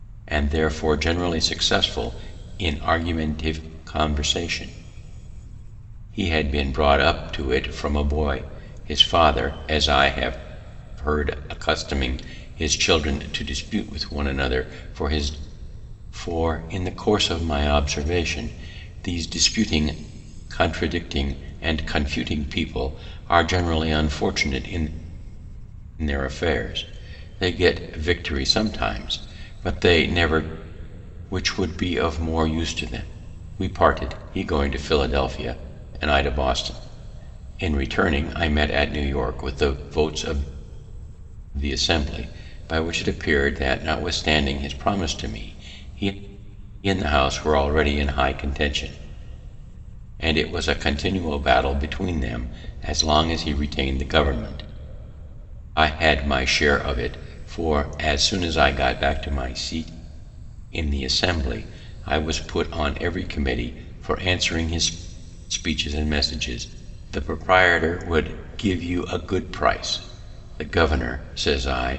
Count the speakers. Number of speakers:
1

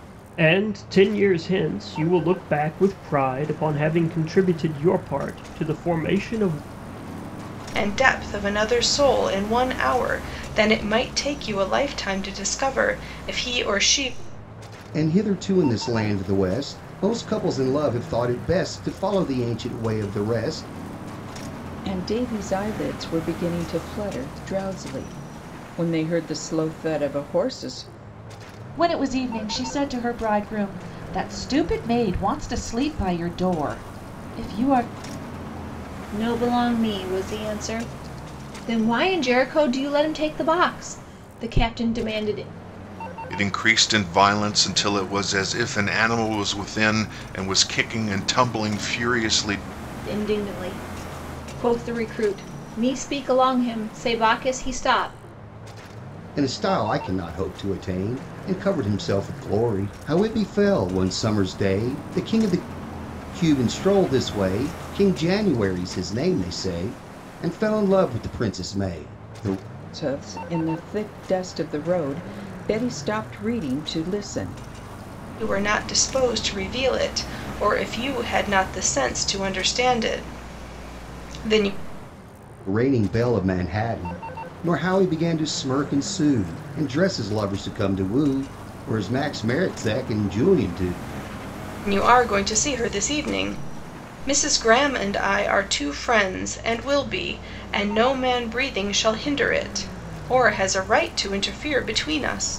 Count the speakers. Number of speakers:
7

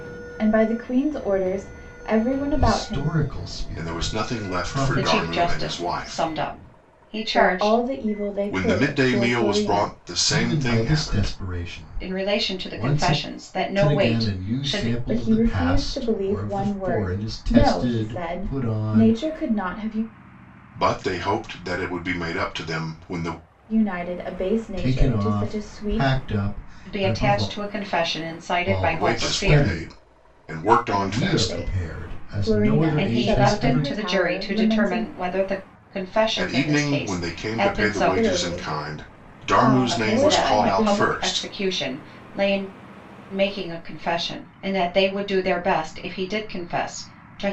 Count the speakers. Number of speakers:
4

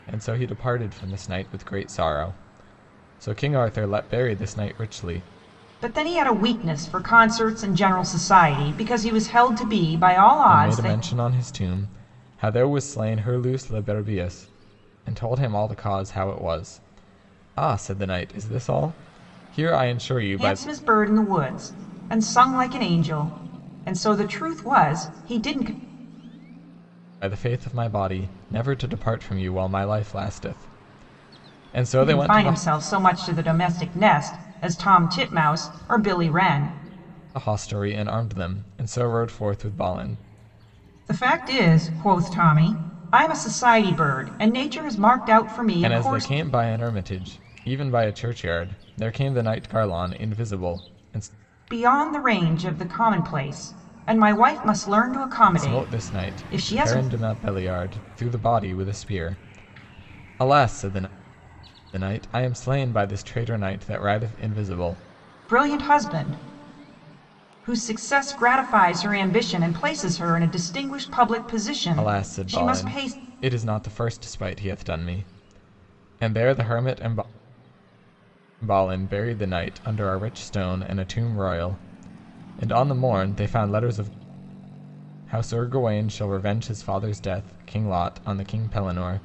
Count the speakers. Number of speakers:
2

